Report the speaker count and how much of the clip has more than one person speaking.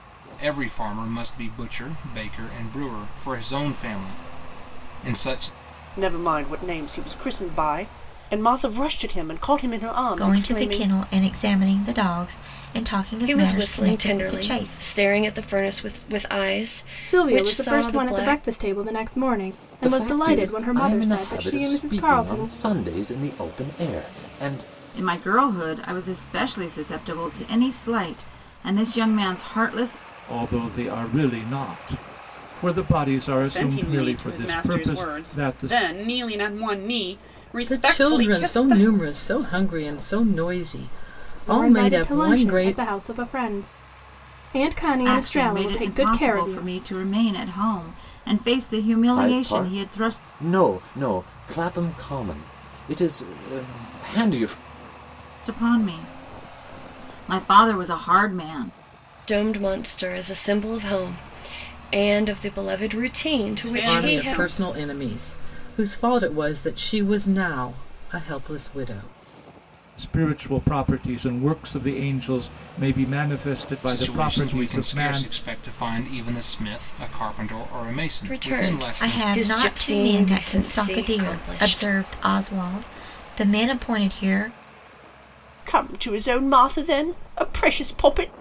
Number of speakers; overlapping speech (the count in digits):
10, about 24%